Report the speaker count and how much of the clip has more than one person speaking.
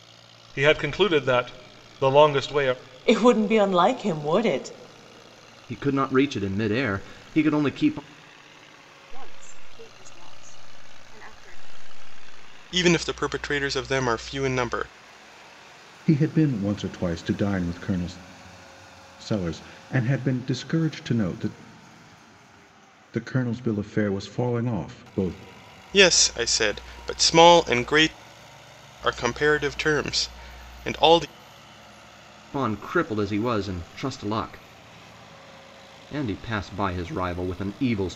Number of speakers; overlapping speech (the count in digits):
6, no overlap